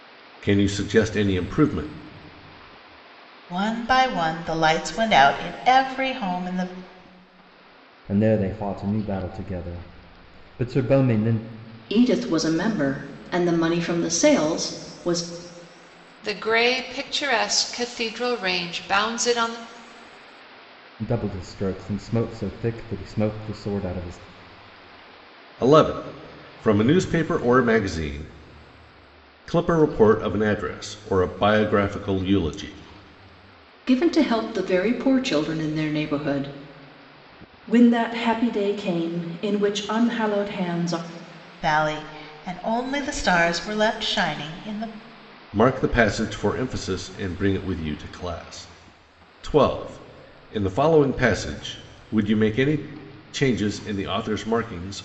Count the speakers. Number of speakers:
five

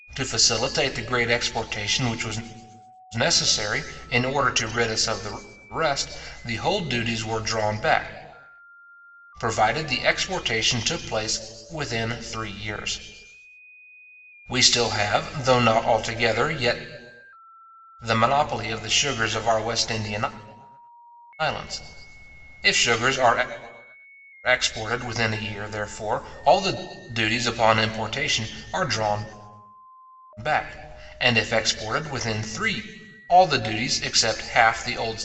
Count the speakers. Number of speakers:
one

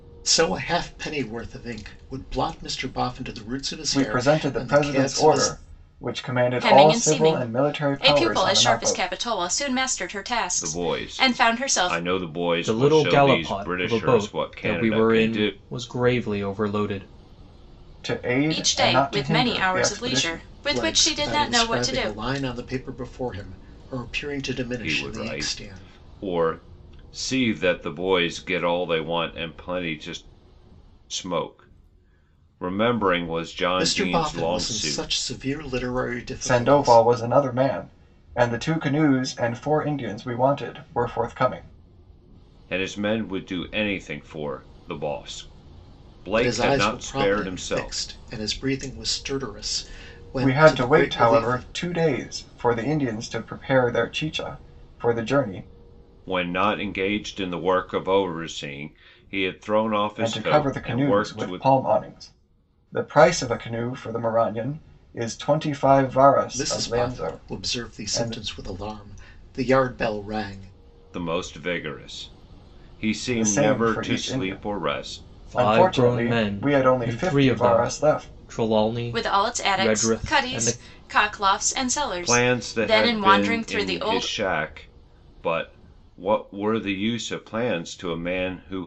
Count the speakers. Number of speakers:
five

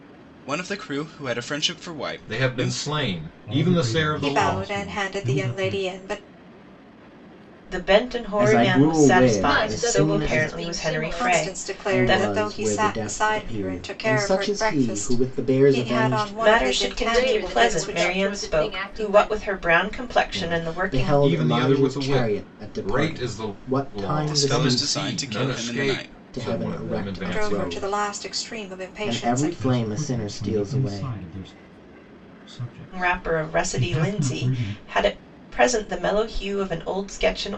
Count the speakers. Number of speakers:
seven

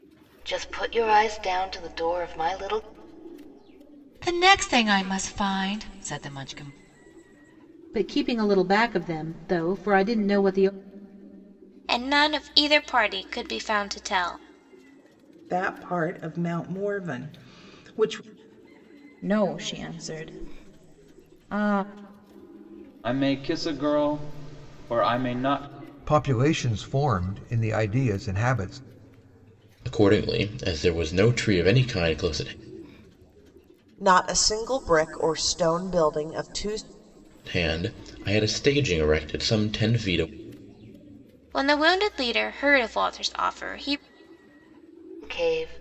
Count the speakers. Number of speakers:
ten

